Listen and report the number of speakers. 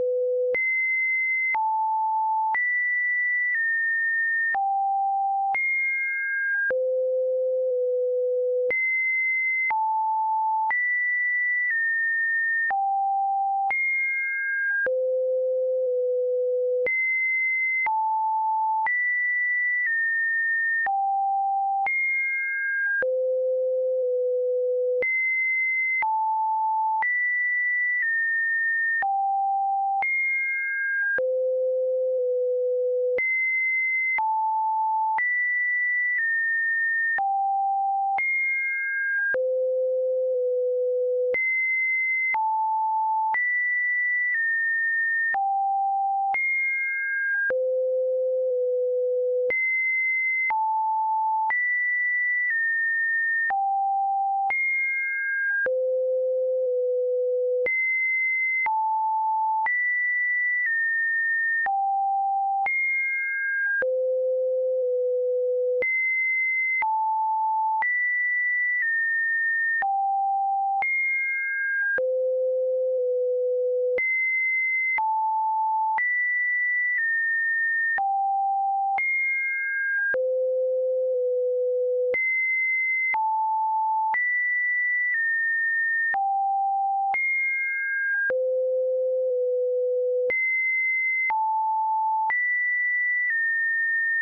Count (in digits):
0